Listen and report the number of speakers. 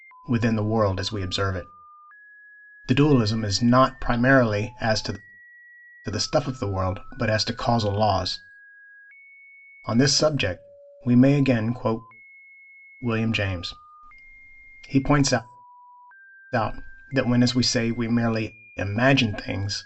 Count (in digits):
1